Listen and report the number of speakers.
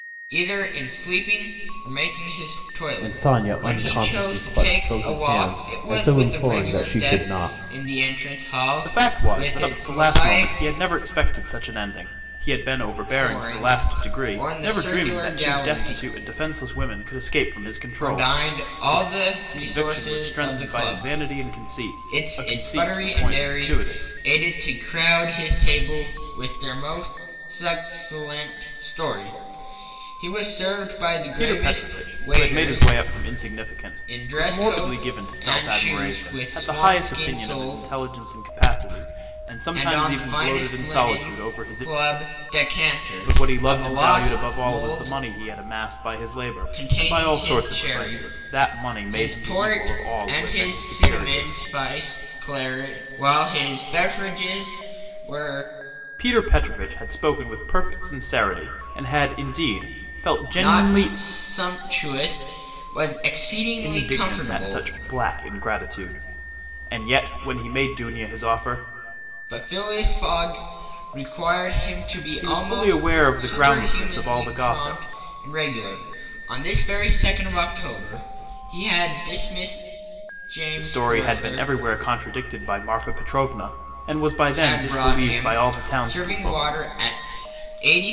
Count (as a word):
two